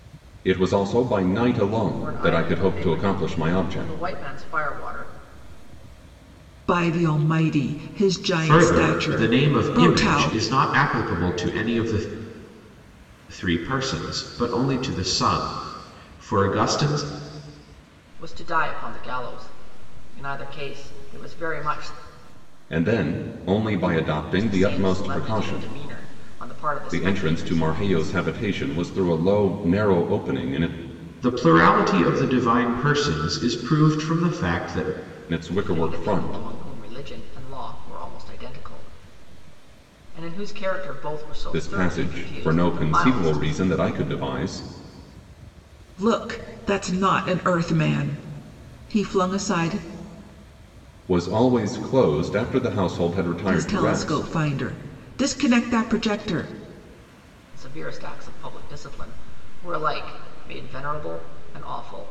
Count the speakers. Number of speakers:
4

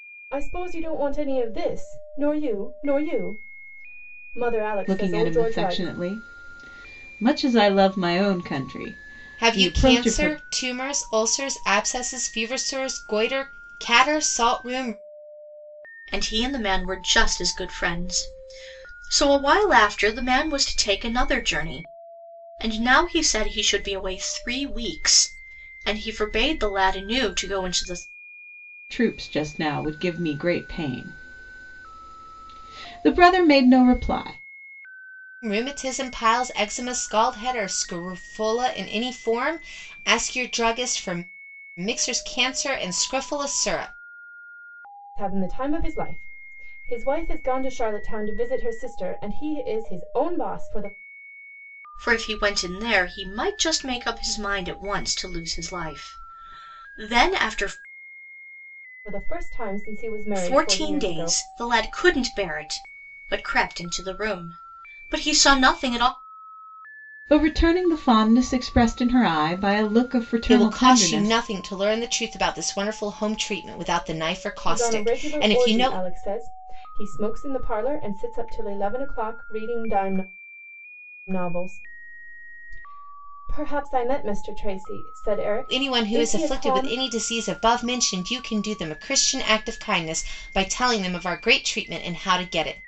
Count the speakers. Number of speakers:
4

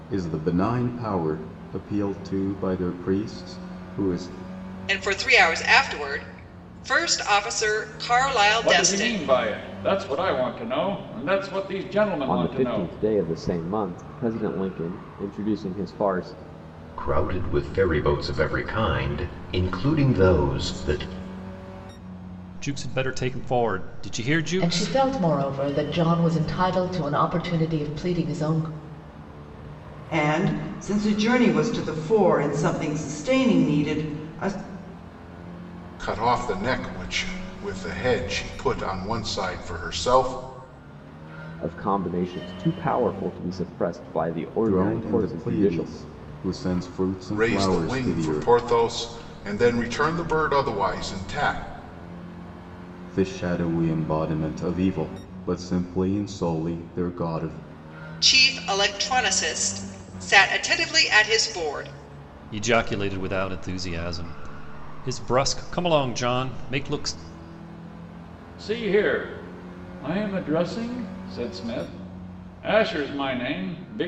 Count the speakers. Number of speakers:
9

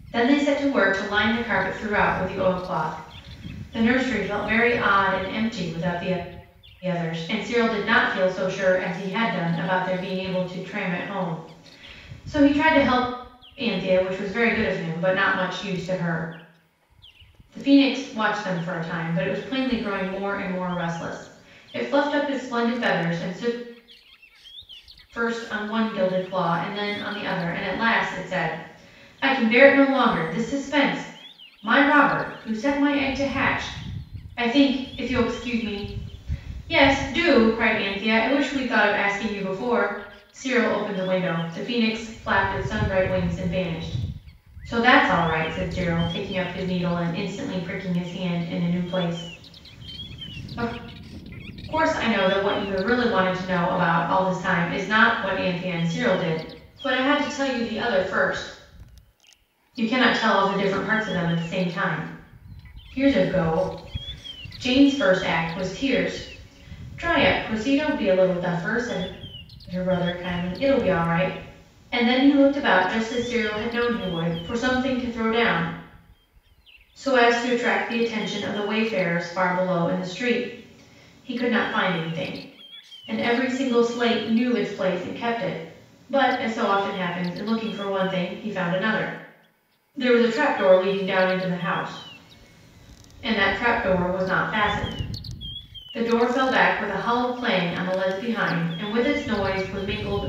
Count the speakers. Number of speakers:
1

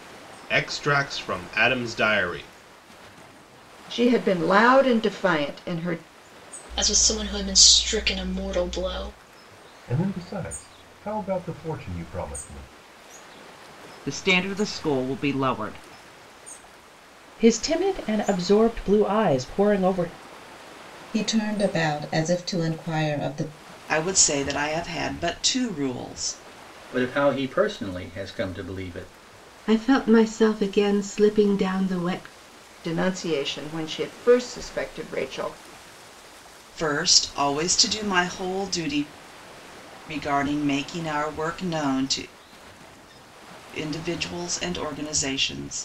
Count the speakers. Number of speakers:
10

